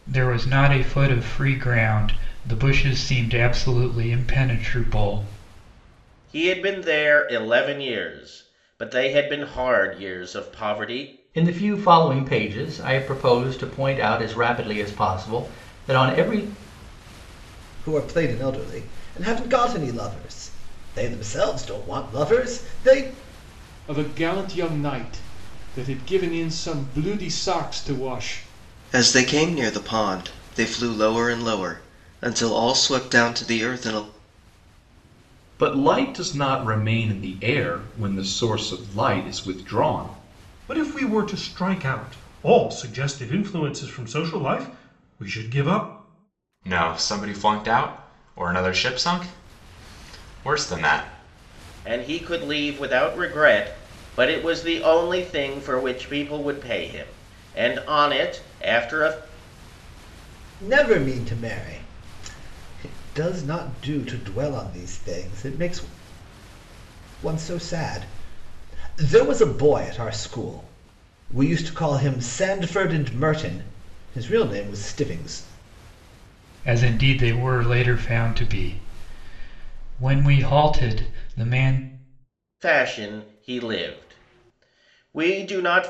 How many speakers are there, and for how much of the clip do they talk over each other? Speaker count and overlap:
nine, no overlap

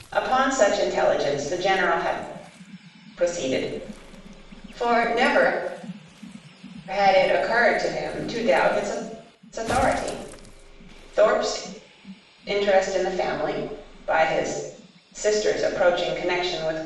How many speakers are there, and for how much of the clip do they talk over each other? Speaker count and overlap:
one, no overlap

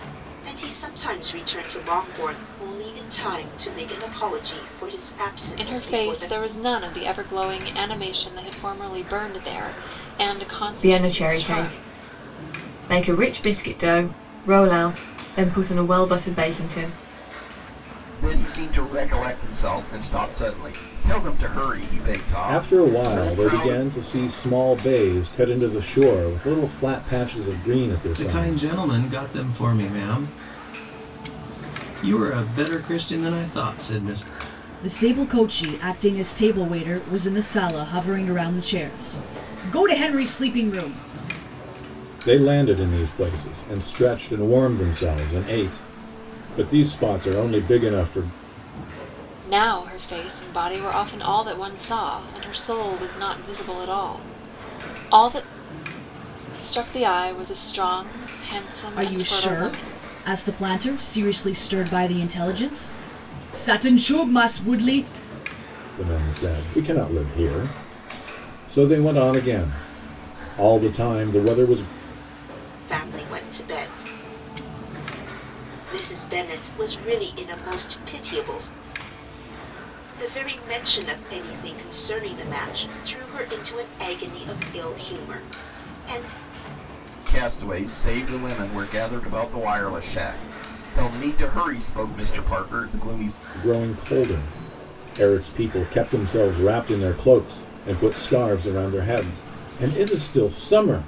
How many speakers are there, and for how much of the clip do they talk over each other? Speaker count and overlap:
seven, about 5%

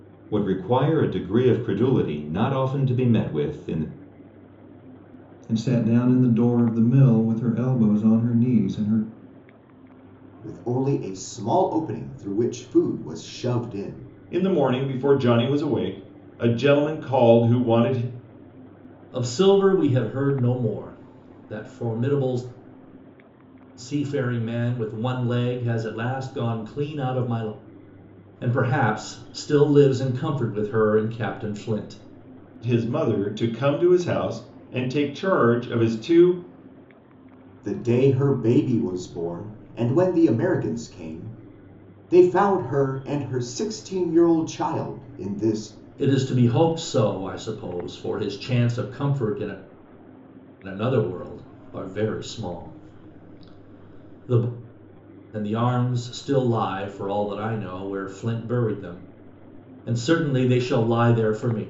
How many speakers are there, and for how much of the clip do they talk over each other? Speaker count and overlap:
five, no overlap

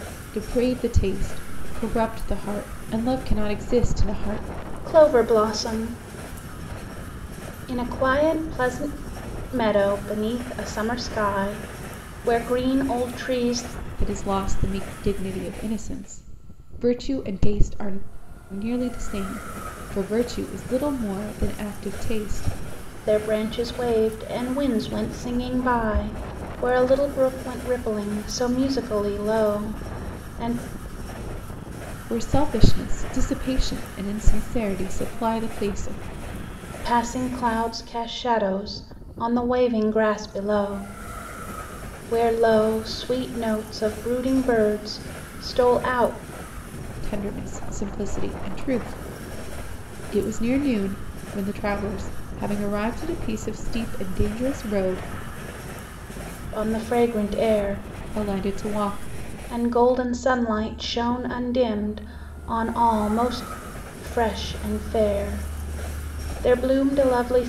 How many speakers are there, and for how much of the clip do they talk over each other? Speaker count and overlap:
two, no overlap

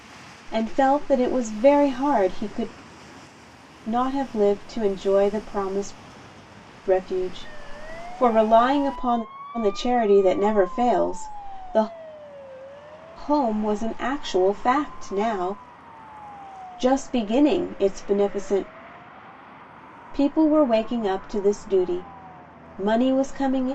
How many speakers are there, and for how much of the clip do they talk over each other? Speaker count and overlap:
one, no overlap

